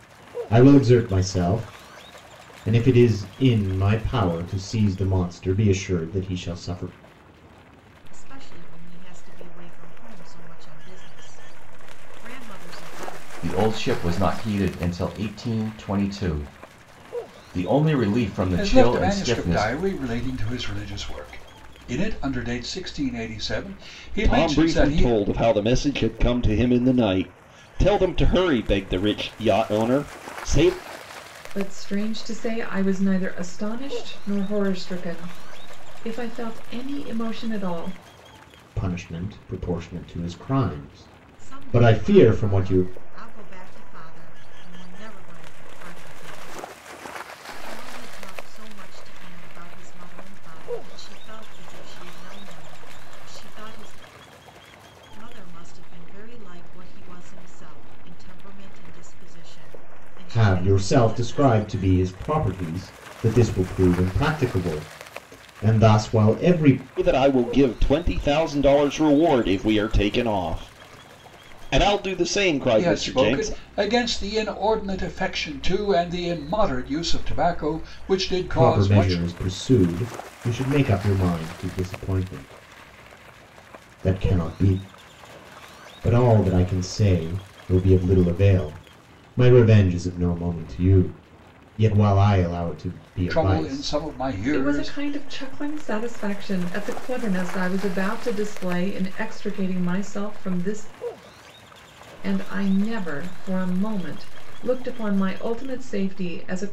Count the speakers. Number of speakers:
six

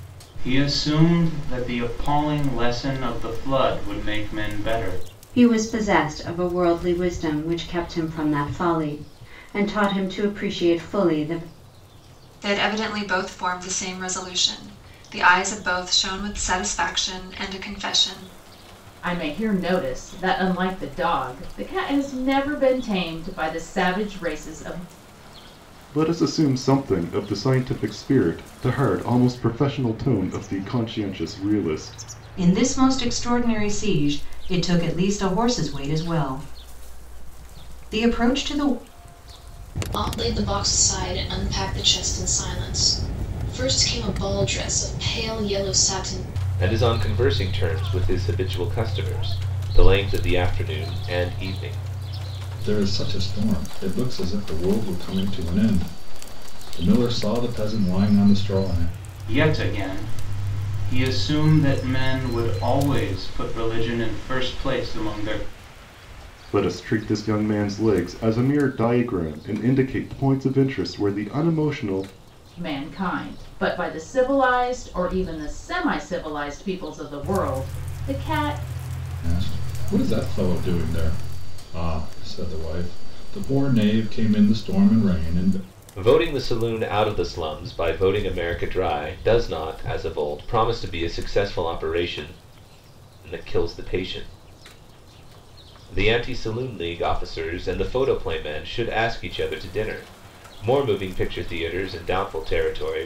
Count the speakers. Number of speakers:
nine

